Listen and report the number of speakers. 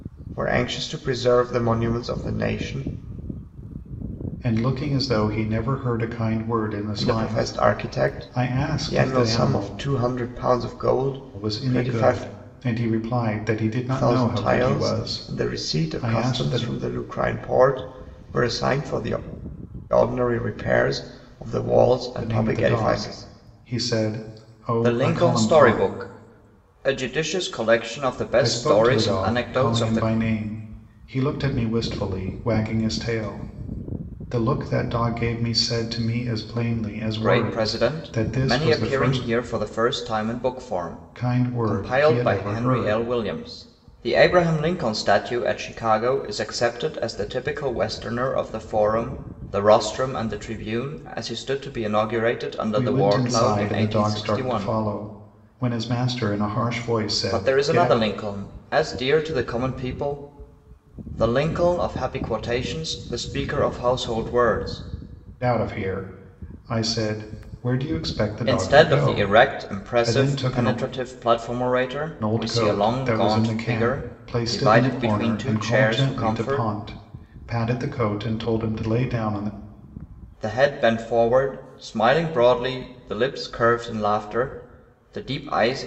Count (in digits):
2